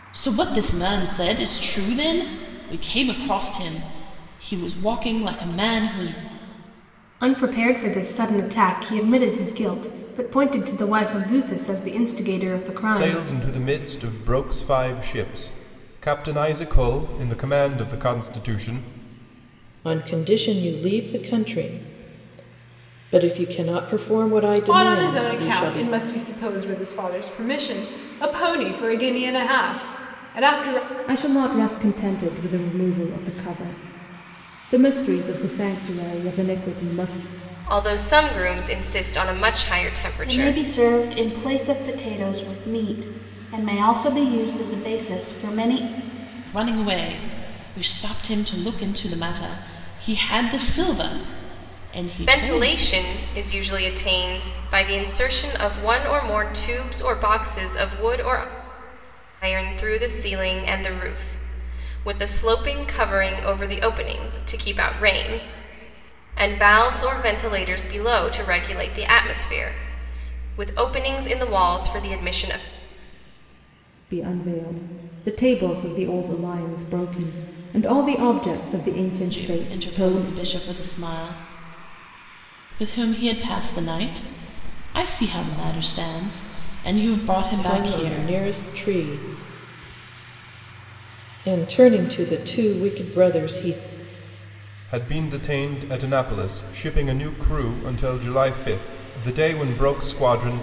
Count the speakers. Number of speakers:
8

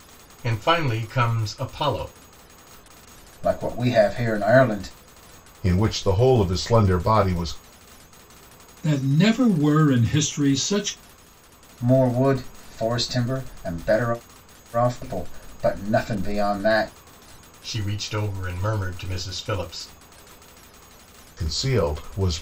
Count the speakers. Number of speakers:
4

